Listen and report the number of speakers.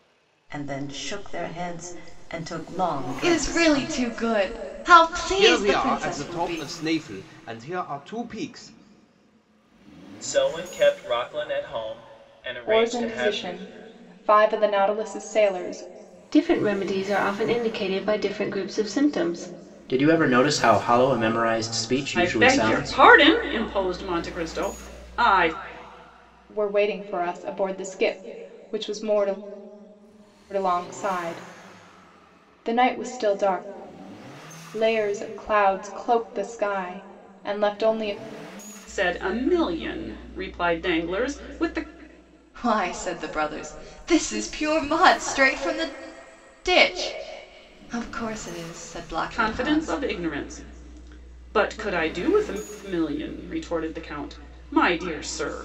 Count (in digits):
8